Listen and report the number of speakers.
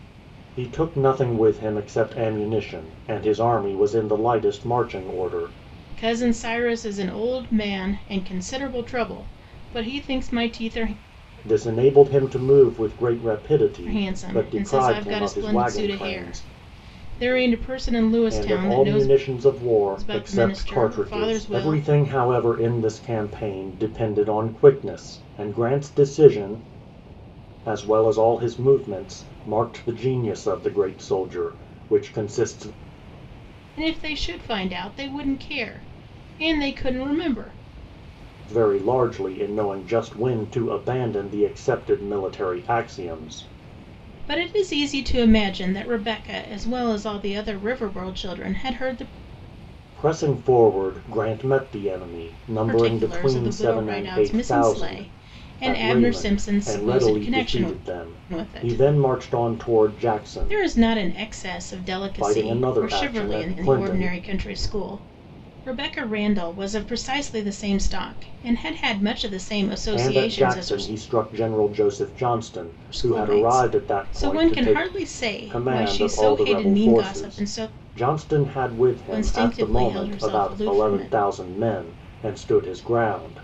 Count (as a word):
two